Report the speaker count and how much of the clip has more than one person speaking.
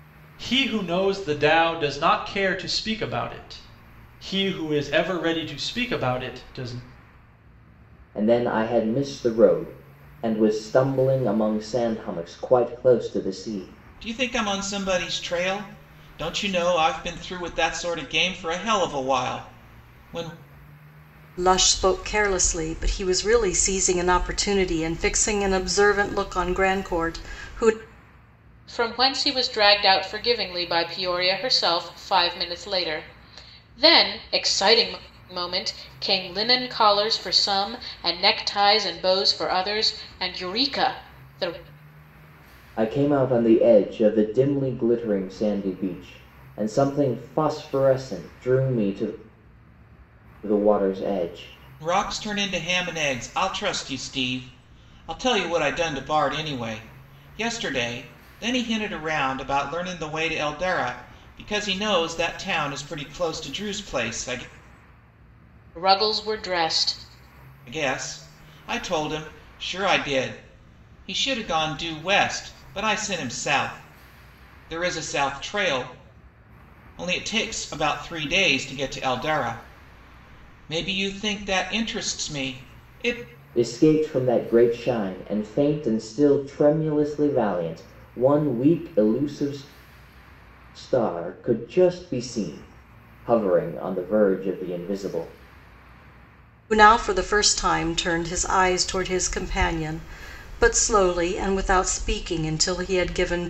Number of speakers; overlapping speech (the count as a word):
five, no overlap